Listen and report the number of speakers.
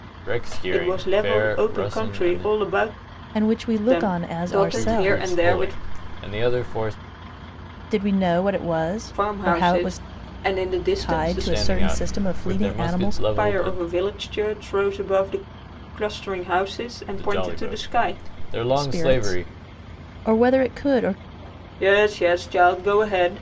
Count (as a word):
three